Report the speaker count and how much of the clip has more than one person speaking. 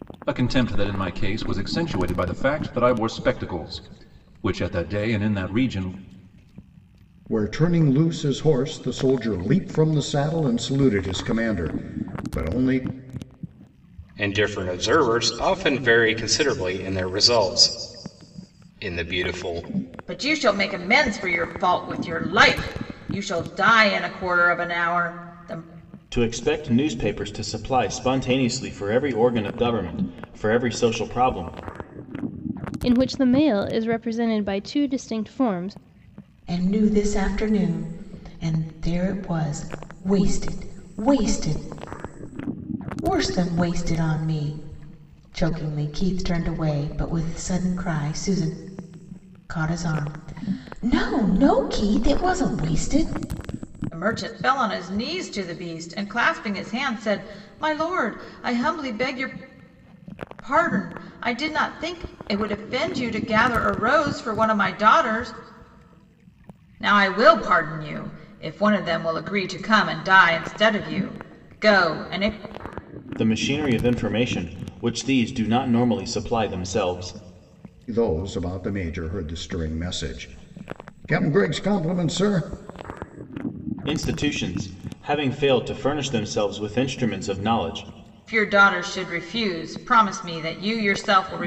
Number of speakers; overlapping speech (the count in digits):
7, no overlap